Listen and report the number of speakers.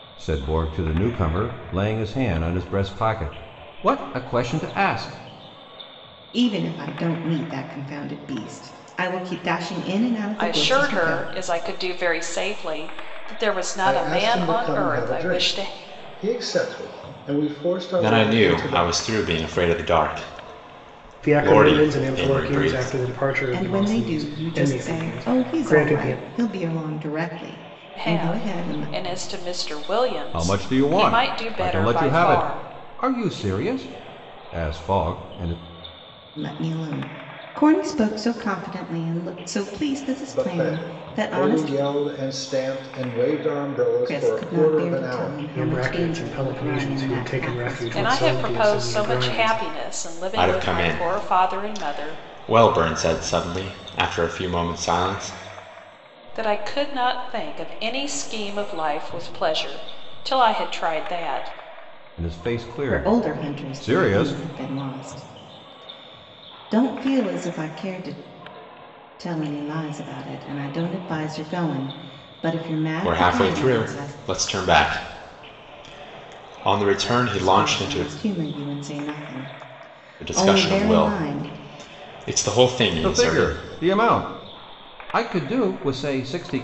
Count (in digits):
6